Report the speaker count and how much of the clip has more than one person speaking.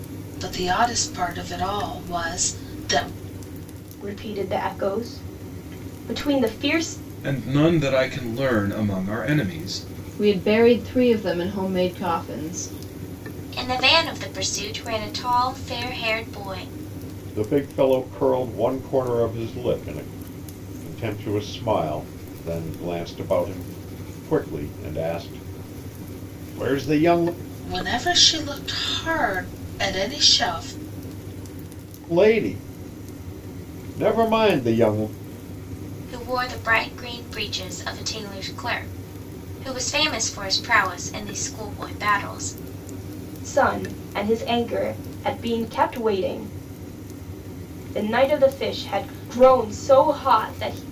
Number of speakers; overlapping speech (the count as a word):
six, no overlap